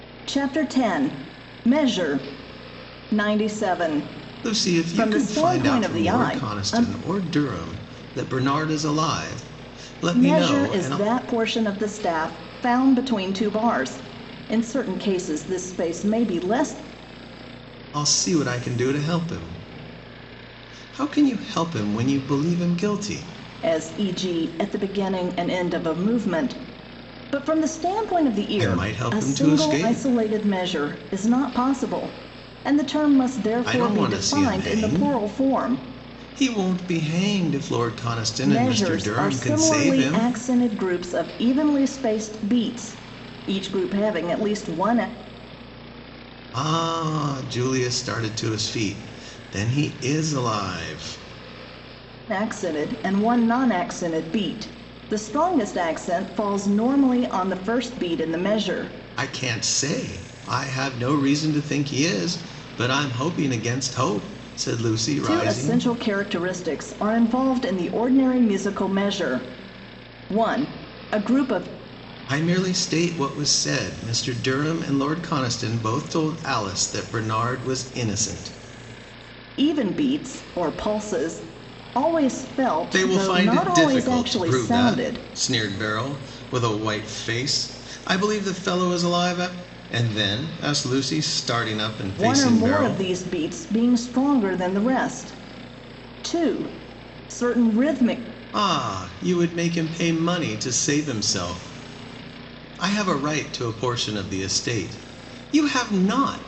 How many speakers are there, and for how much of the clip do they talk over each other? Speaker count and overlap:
2, about 12%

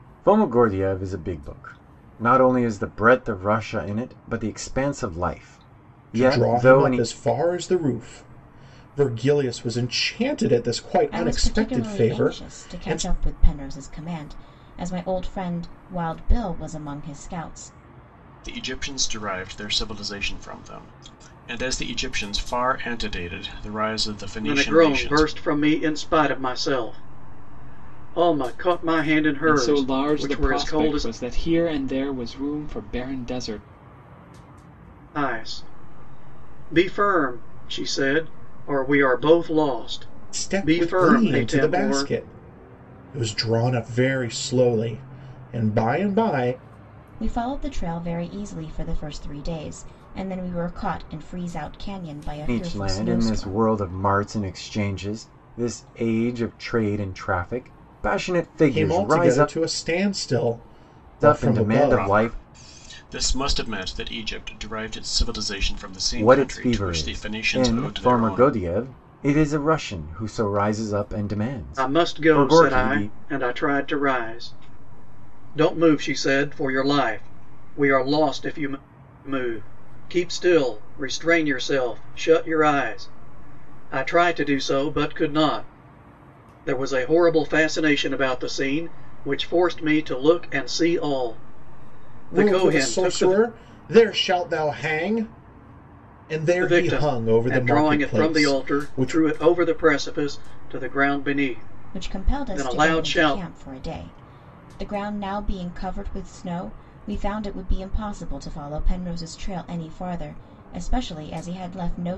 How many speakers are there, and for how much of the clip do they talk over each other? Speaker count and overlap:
6, about 17%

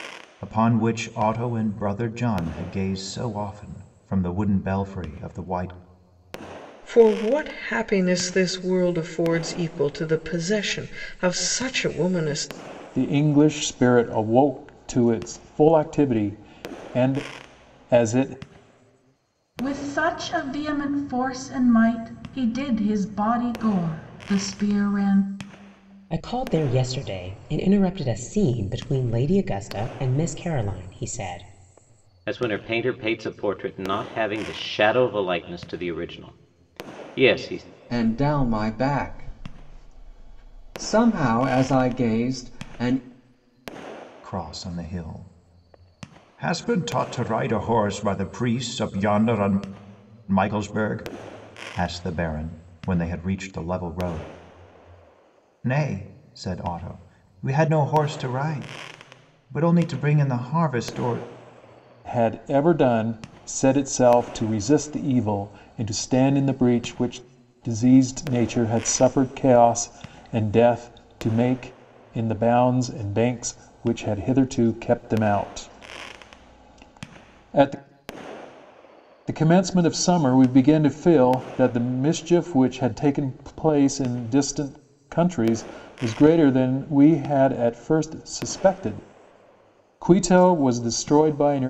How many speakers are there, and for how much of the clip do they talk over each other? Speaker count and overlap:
7, no overlap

